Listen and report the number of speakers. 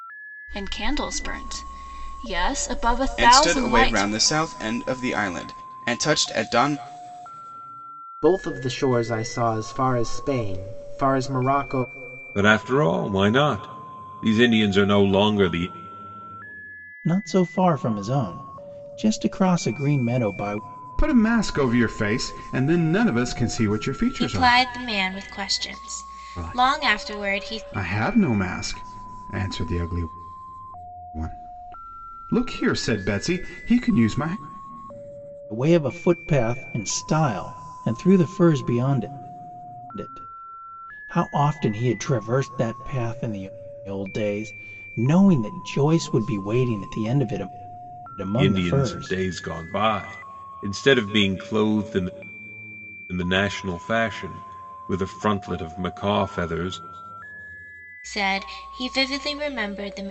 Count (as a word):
seven